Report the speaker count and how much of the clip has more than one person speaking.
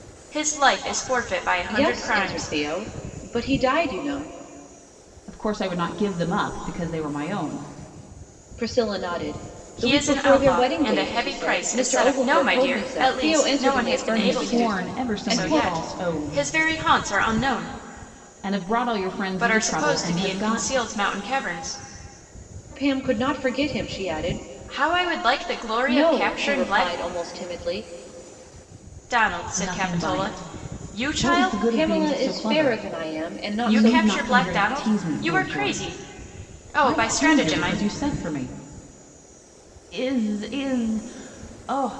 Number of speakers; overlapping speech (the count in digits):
3, about 43%